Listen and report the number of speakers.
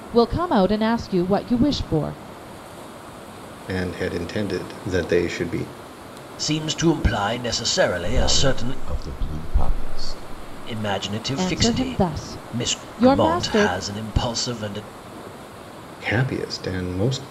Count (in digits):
4